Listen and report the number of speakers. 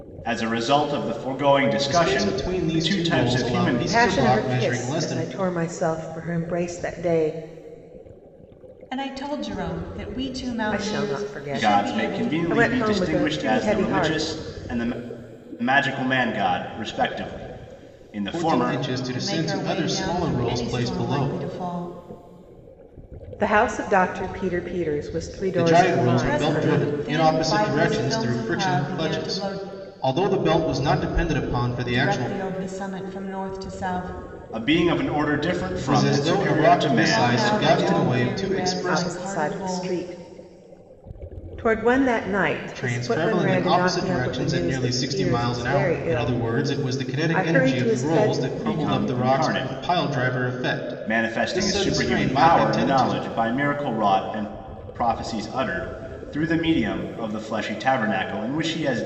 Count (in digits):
4